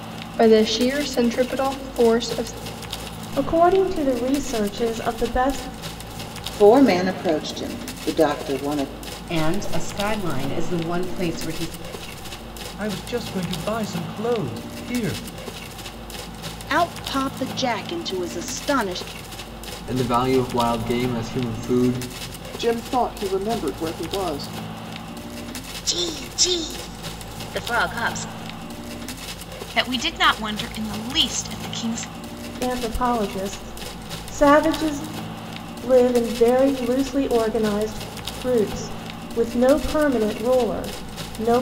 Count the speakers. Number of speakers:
10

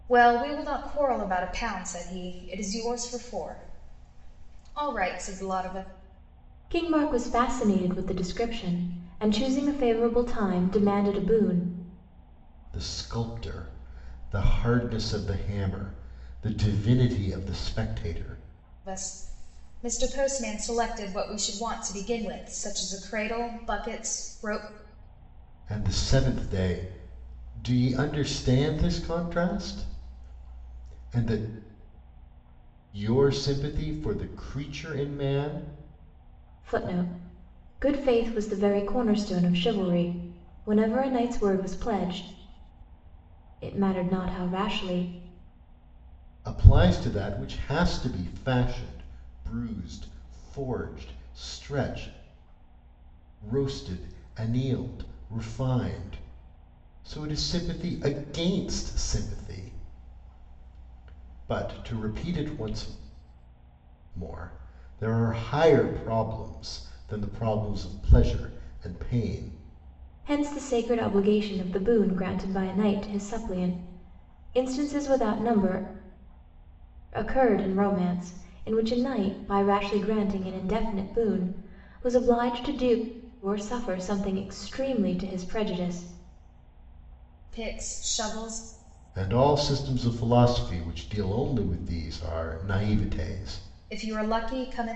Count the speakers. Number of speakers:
3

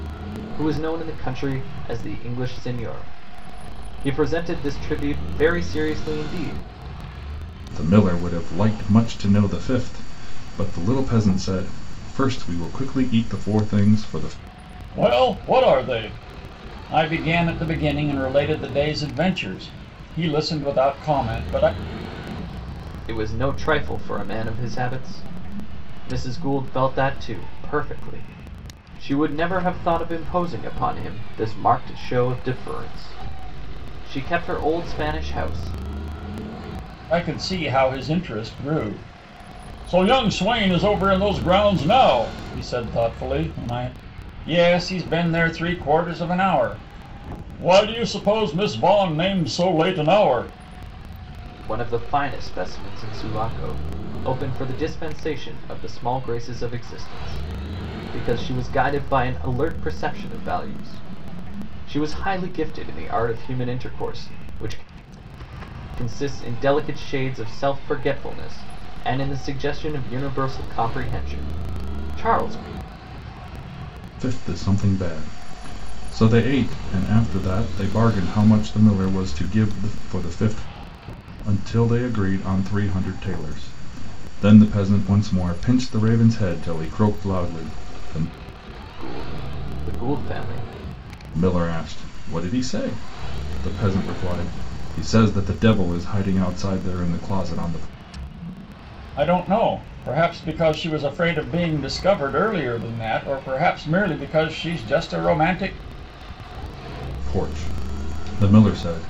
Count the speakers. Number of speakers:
3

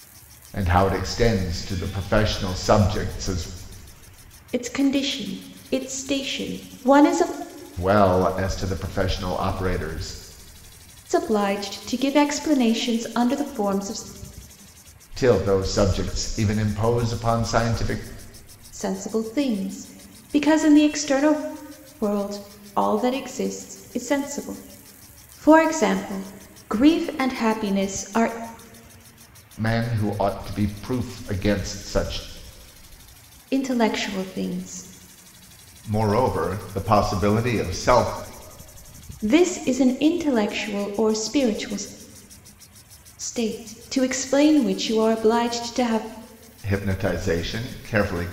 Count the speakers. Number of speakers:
2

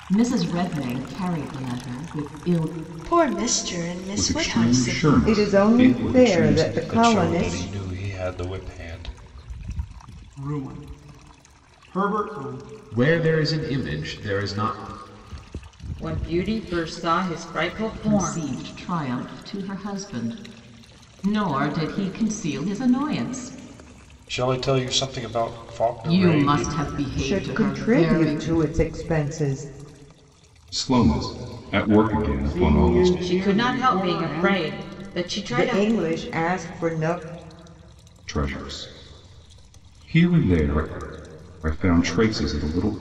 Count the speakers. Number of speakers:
8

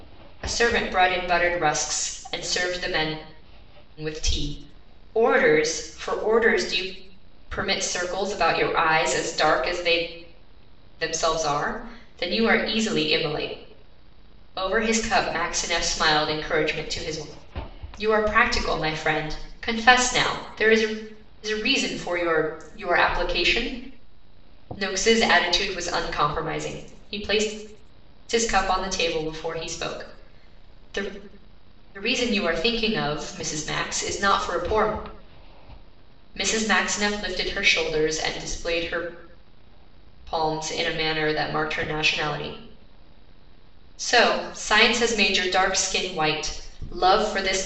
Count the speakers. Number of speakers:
1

